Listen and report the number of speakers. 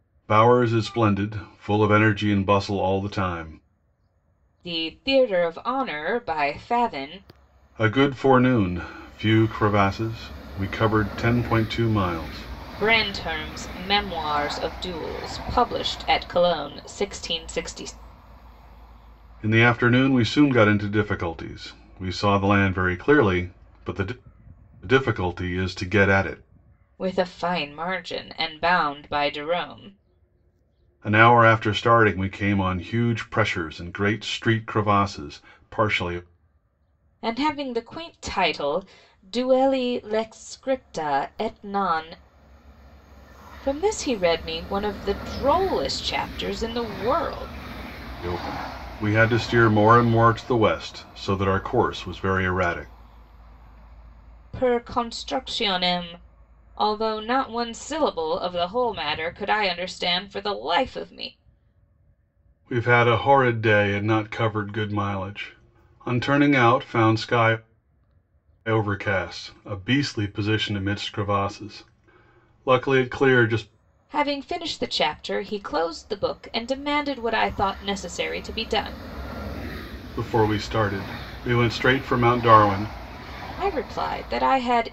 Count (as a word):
two